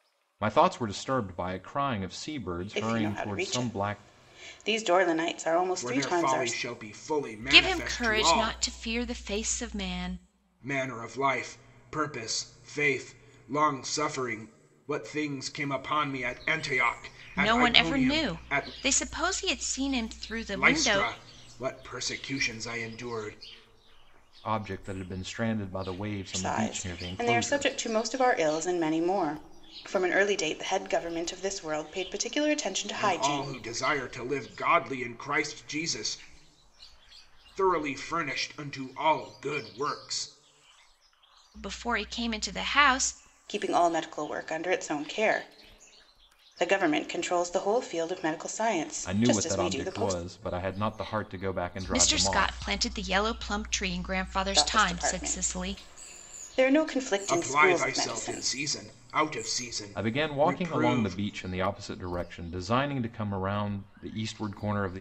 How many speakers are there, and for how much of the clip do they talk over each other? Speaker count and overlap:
four, about 20%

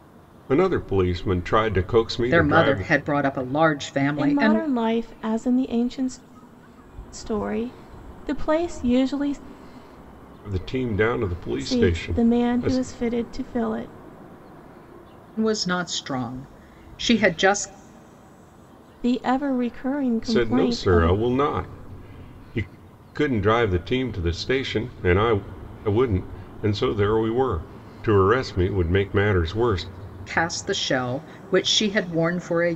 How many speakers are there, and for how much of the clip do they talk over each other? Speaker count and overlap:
three, about 10%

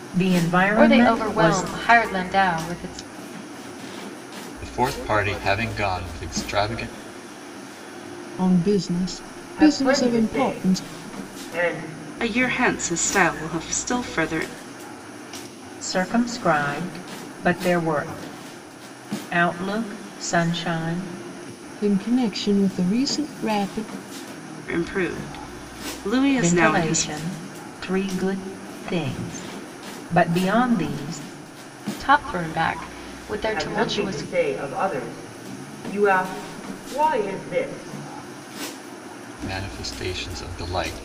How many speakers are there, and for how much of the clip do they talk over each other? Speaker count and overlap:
six, about 10%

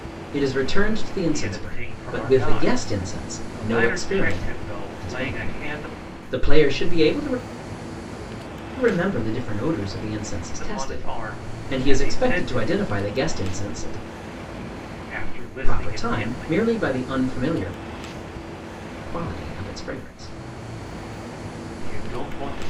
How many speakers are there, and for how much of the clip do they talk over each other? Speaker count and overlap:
two, about 28%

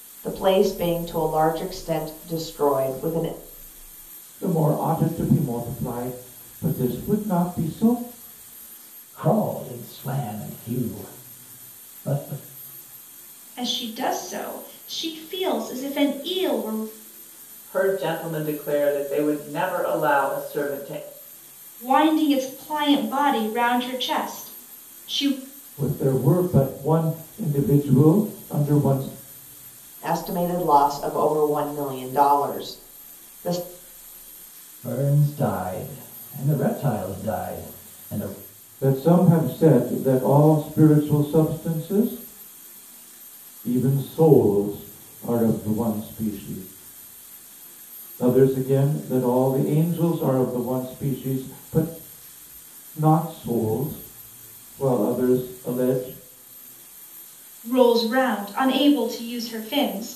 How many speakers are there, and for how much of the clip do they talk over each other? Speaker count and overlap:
five, no overlap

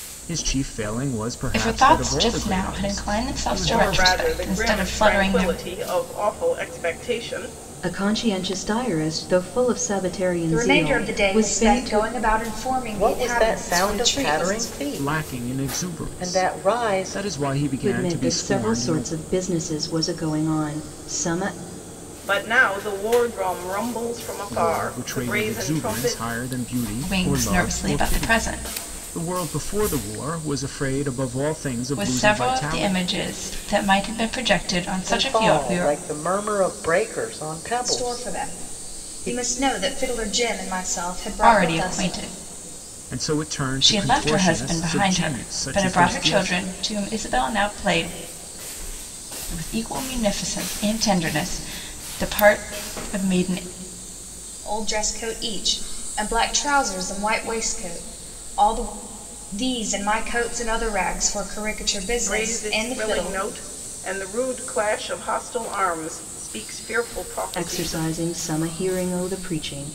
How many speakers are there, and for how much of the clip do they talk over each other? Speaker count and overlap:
six, about 33%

